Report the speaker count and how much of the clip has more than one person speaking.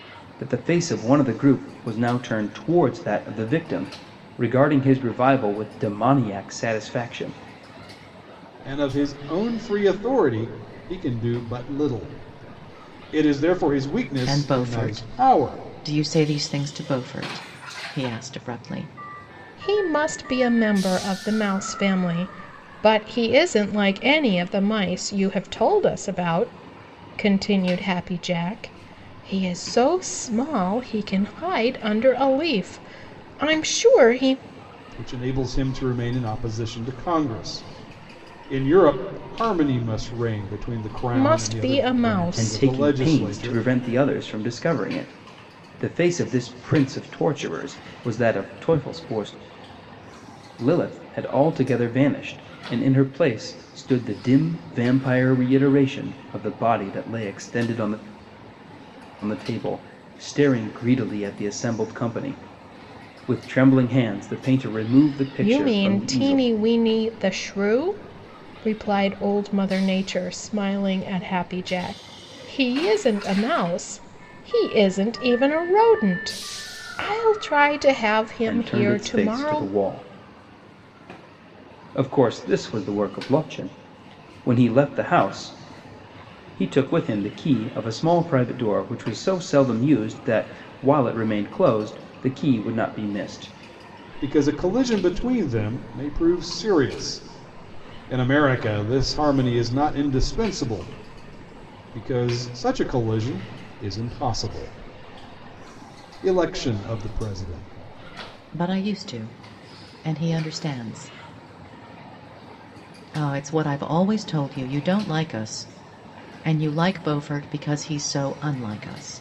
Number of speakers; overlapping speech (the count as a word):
four, about 5%